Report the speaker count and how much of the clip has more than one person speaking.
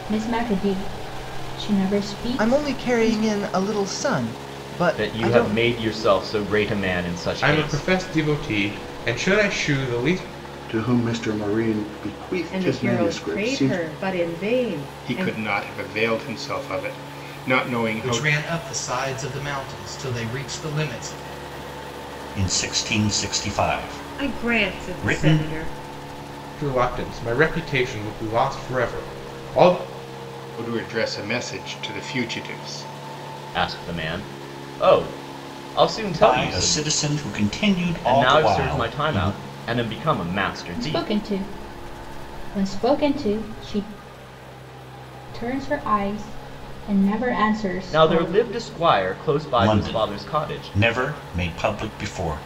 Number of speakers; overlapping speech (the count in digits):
10, about 18%